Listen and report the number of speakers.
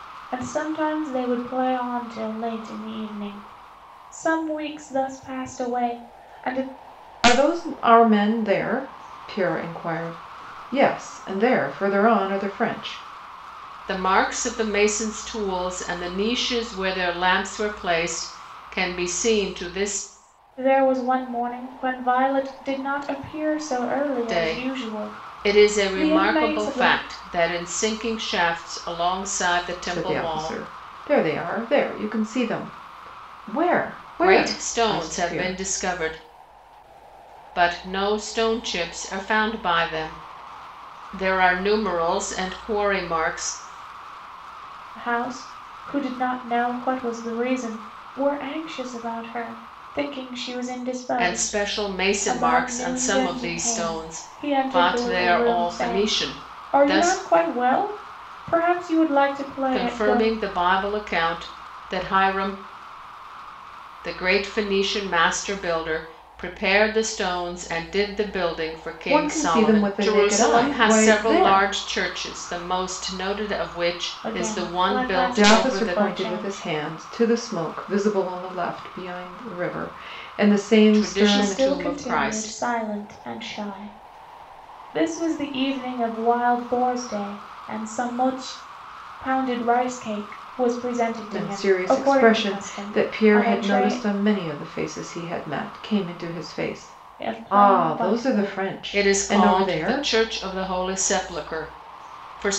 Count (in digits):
3